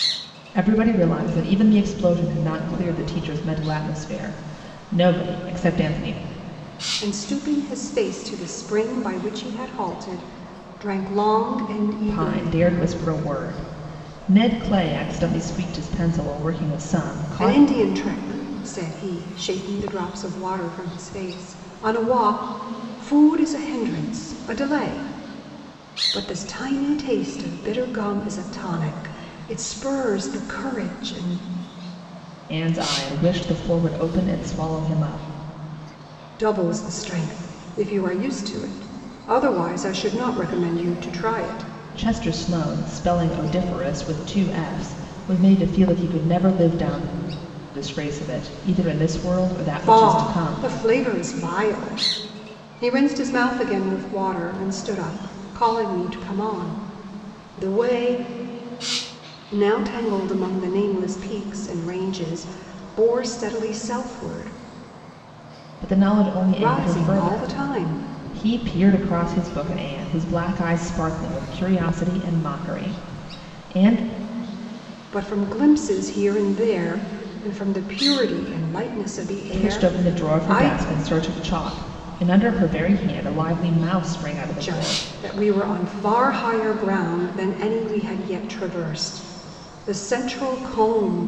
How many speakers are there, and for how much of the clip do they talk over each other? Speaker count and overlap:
2, about 5%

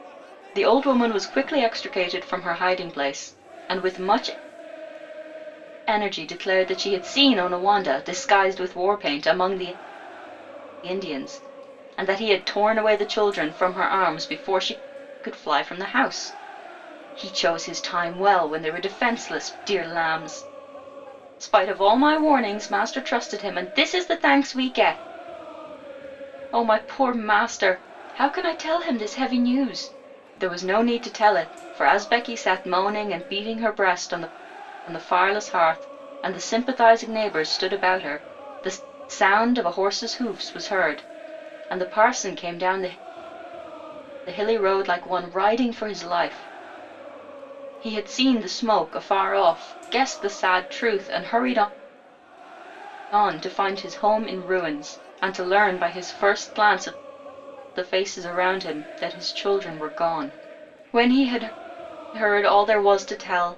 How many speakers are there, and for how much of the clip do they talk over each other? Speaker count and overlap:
1, no overlap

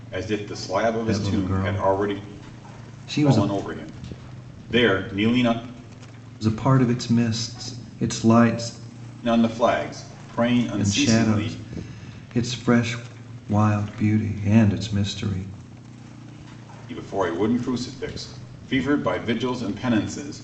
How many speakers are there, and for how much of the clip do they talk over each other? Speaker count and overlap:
2, about 11%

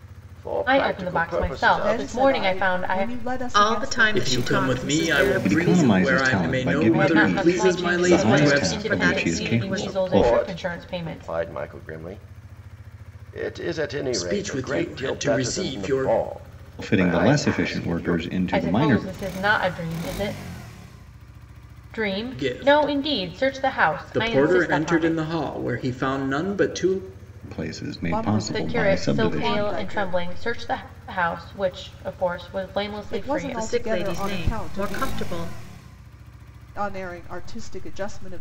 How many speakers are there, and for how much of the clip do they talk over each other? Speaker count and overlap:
6, about 55%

